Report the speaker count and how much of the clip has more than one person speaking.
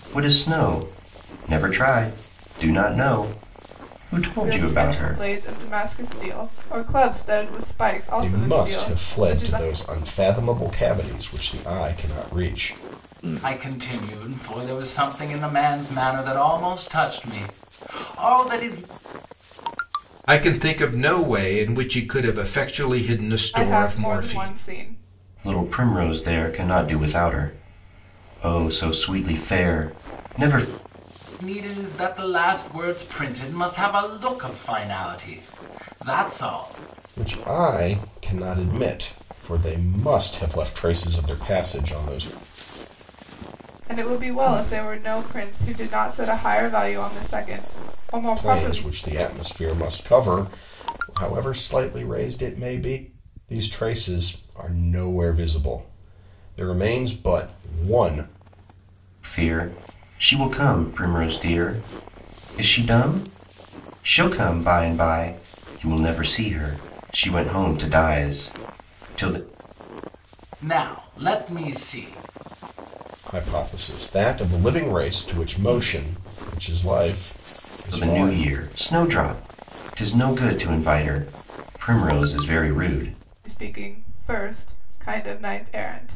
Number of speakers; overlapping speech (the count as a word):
five, about 5%